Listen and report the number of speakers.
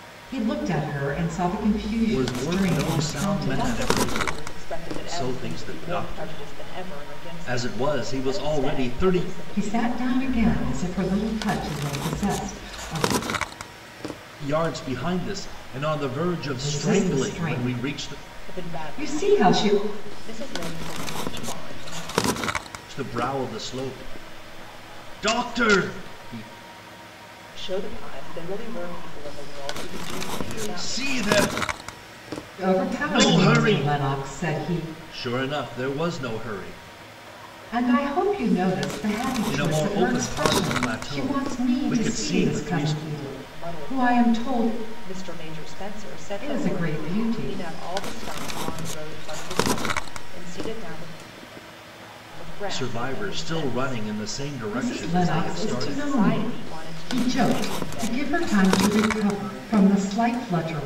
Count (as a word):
three